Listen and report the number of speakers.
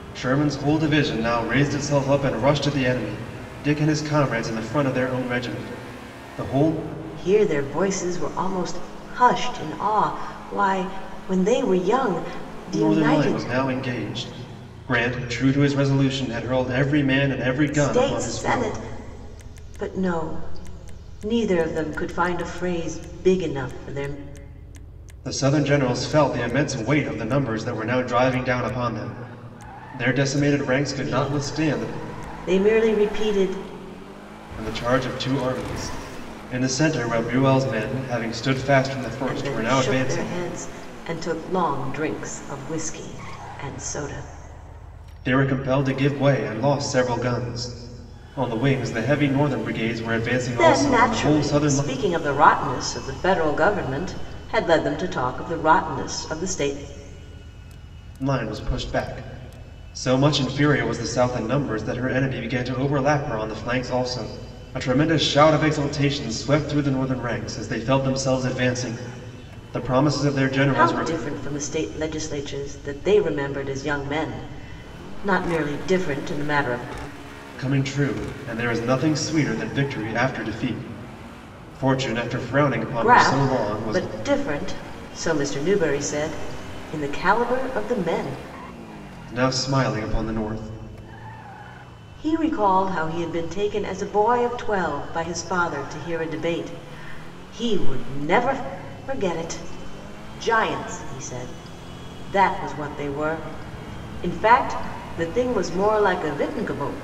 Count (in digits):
2